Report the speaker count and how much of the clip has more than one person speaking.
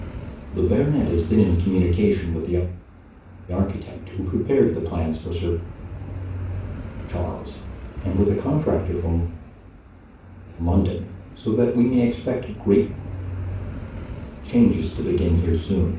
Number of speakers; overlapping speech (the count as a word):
one, no overlap